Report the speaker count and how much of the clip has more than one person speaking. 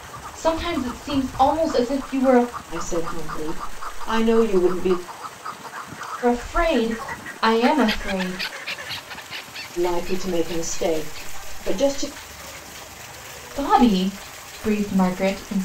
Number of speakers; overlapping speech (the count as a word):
two, no overlap